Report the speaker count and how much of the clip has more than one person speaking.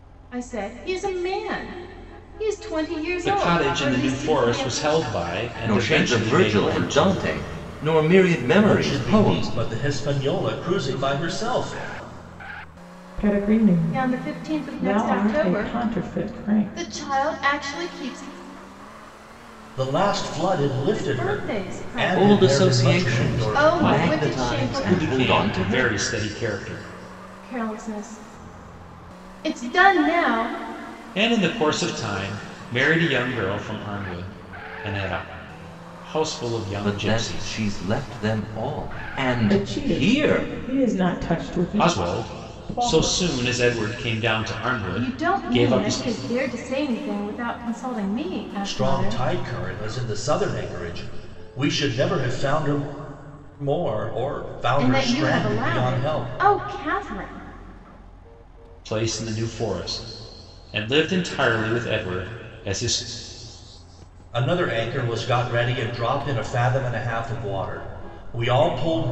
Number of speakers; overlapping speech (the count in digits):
5, about 27%